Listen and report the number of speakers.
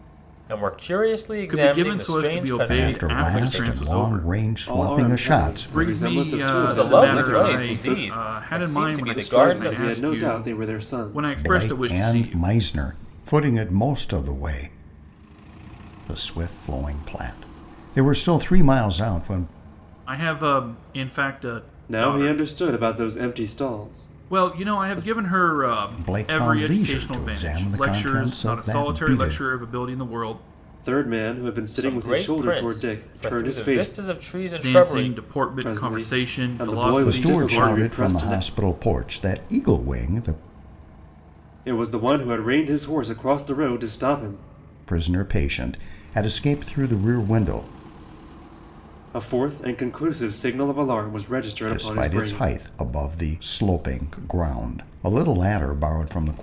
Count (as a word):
four